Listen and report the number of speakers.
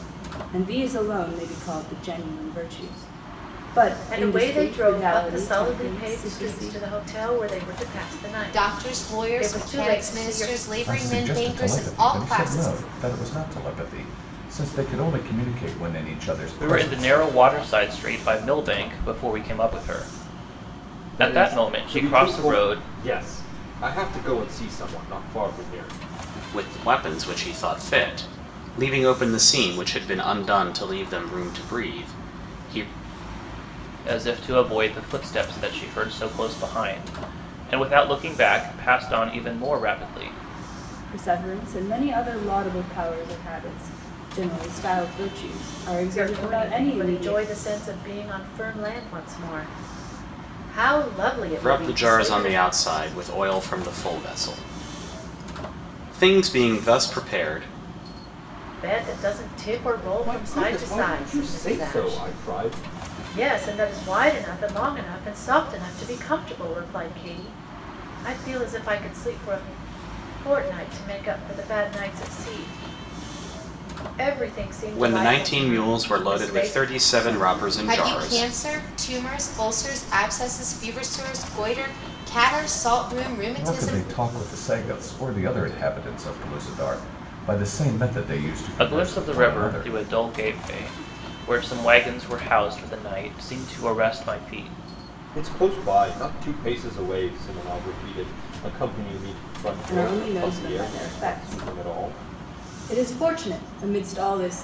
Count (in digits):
7